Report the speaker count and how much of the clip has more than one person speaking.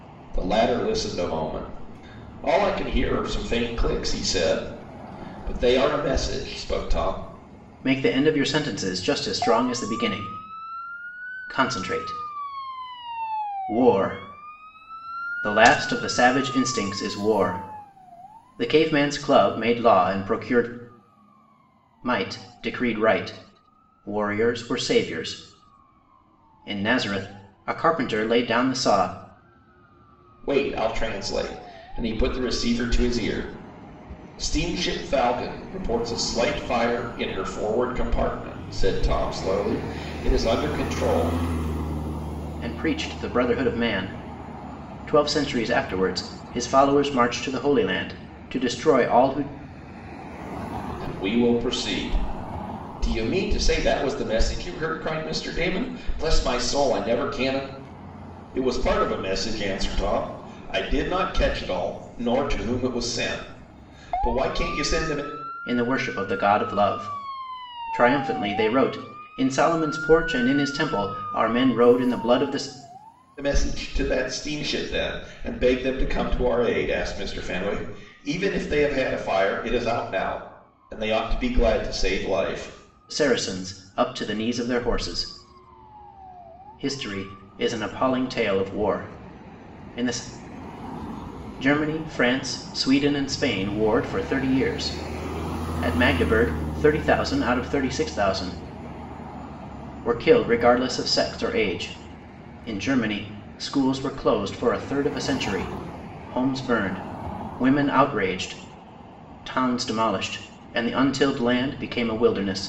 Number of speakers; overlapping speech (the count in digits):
2, no overlap